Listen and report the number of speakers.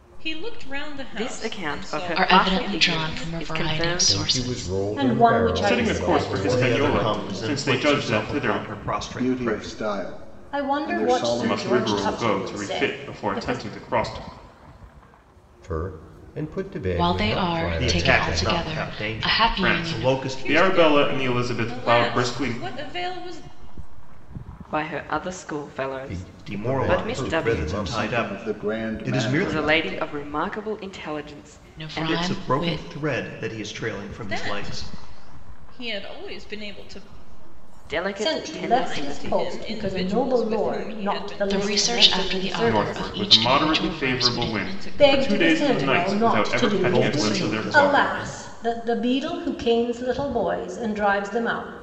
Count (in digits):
8